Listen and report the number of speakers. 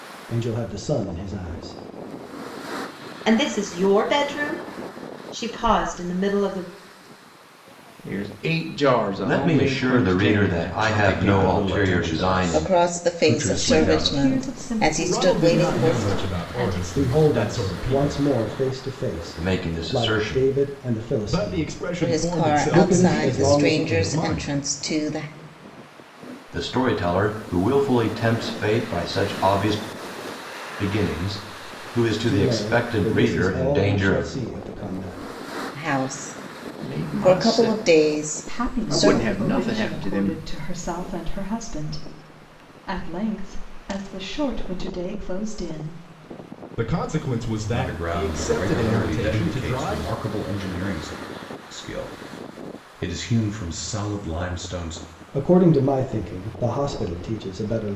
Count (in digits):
8